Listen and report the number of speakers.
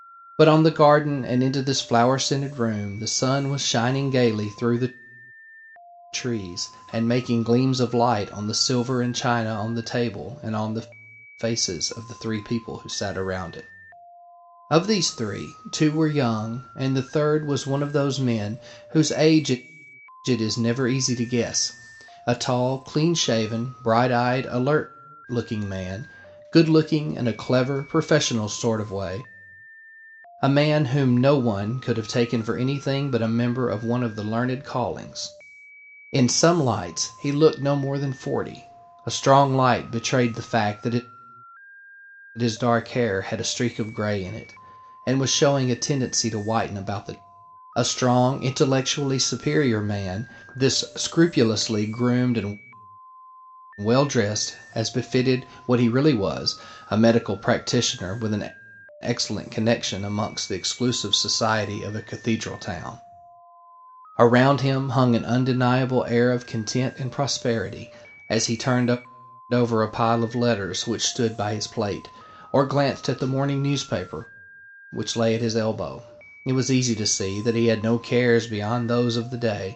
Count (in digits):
1